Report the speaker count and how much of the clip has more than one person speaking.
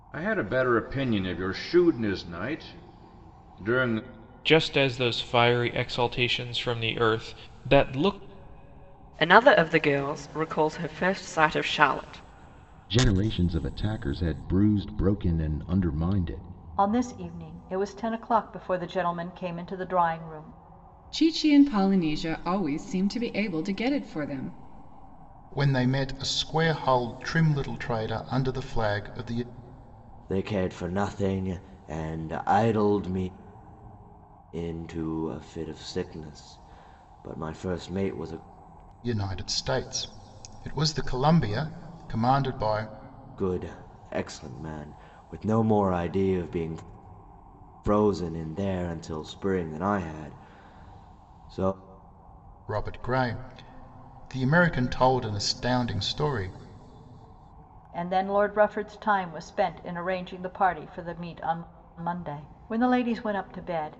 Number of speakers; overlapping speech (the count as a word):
eight, no overlap